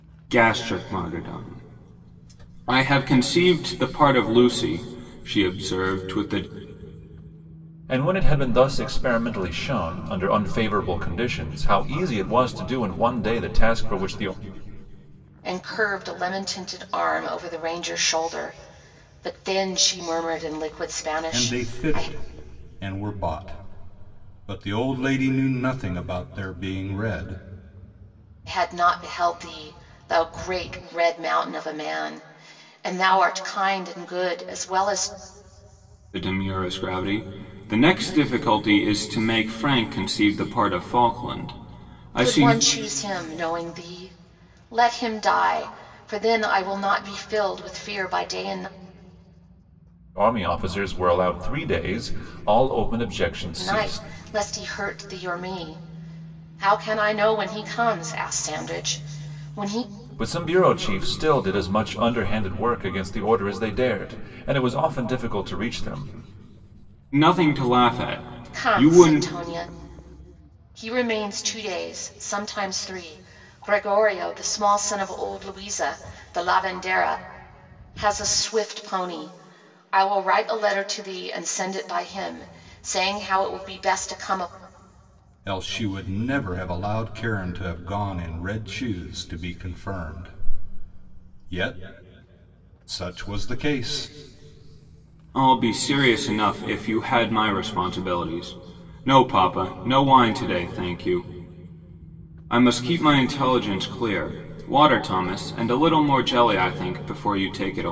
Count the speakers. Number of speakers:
four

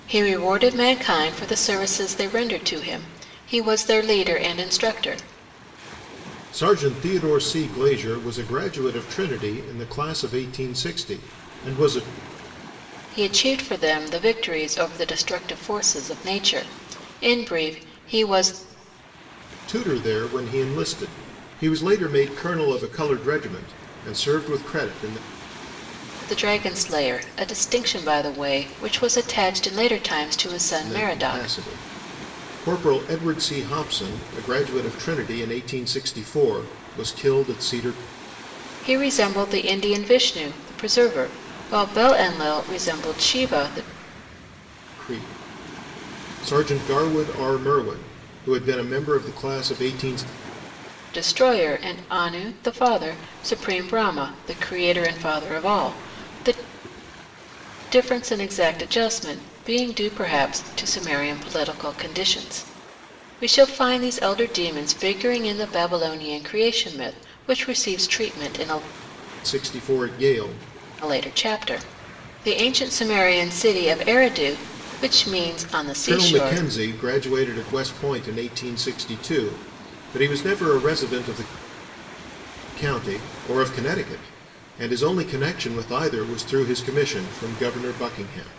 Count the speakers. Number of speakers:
two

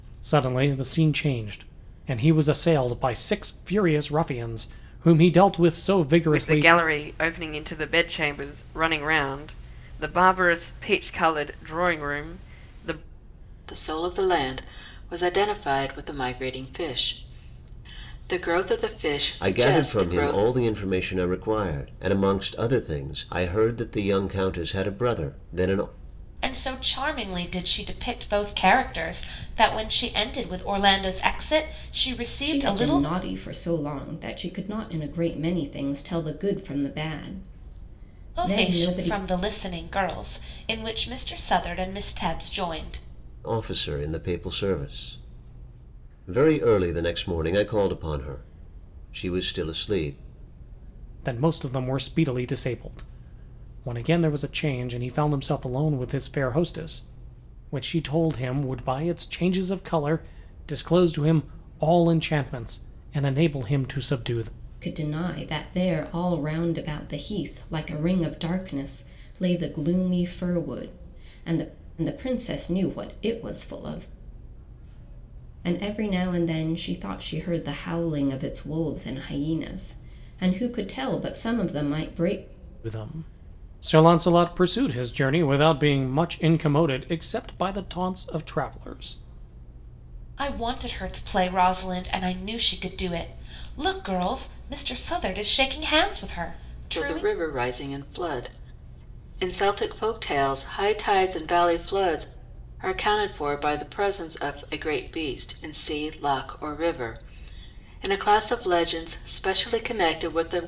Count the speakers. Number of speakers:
six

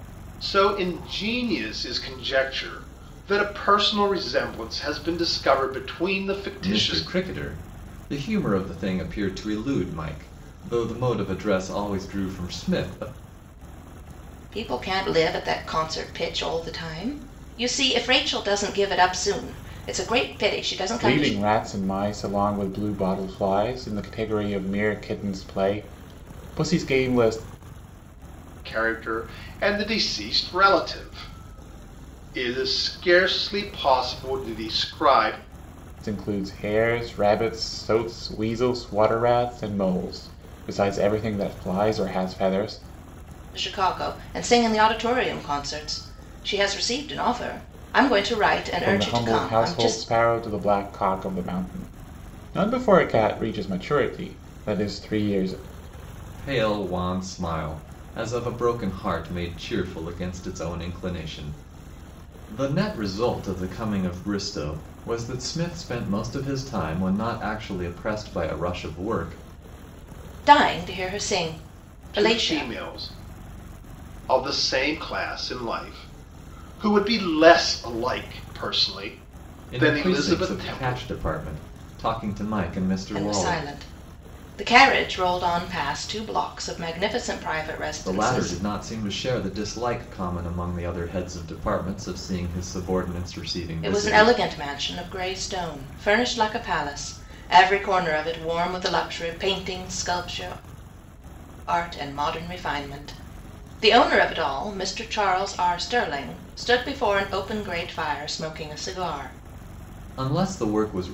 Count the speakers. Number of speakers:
four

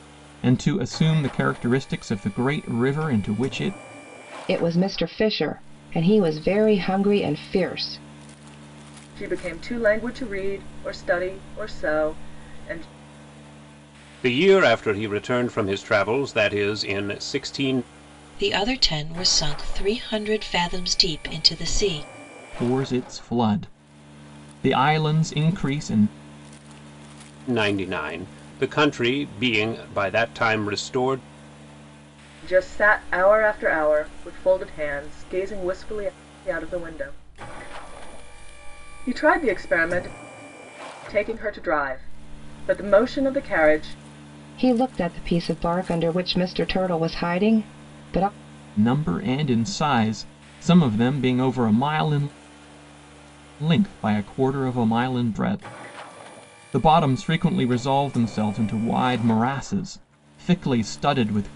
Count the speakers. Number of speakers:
five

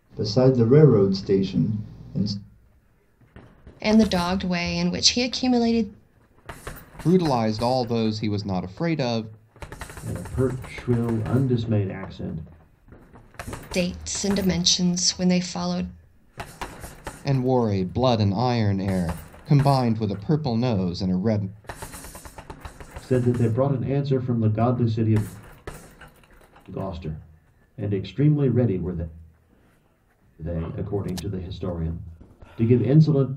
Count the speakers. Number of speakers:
four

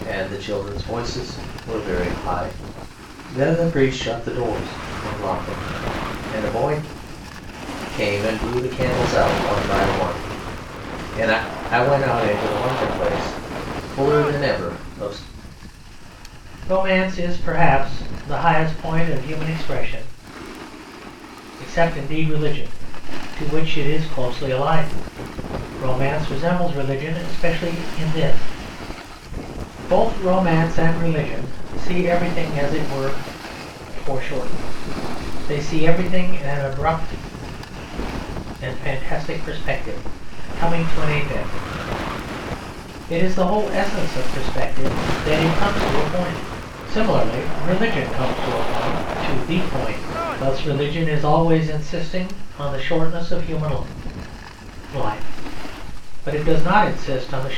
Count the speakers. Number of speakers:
one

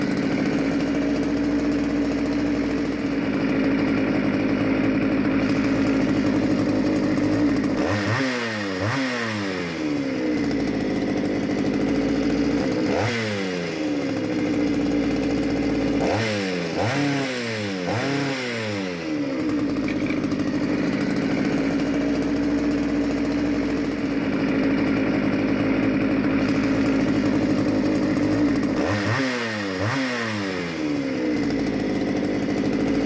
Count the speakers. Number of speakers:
zero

